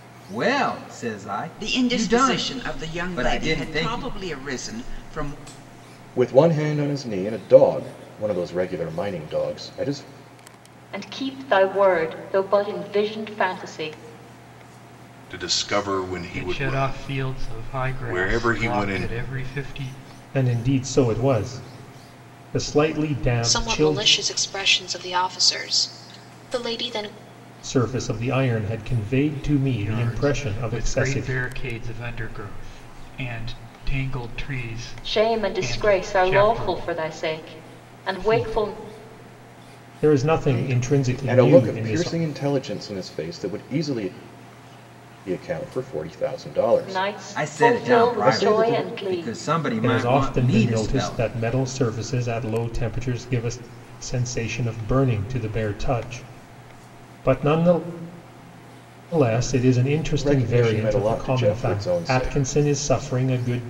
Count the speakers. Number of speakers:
8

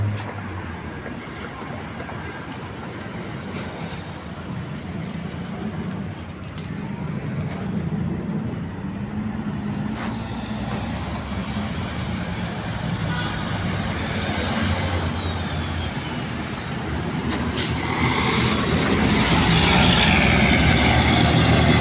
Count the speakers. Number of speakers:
0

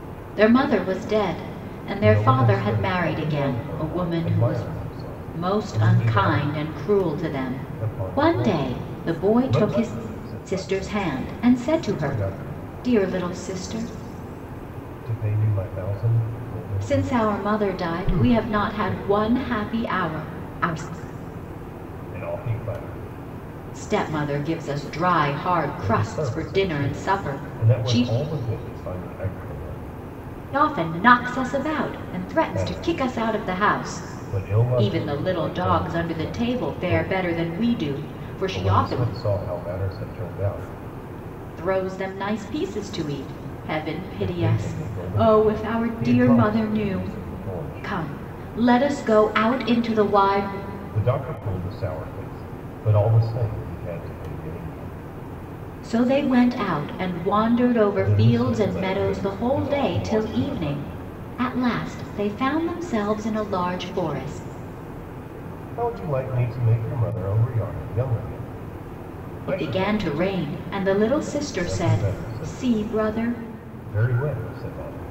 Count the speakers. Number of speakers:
2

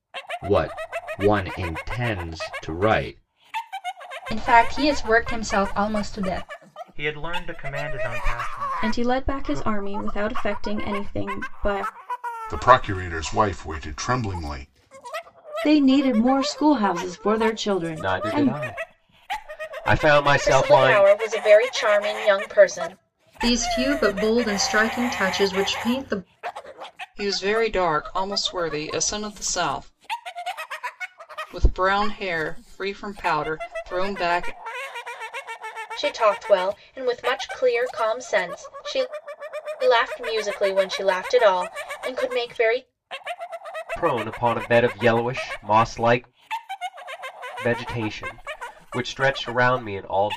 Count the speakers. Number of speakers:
10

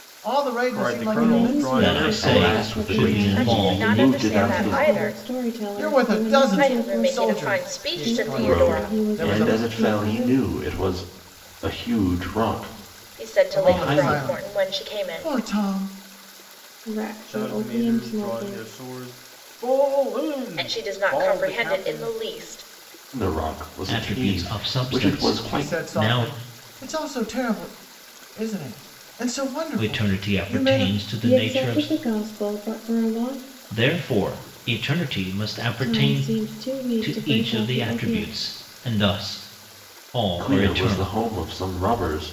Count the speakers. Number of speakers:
6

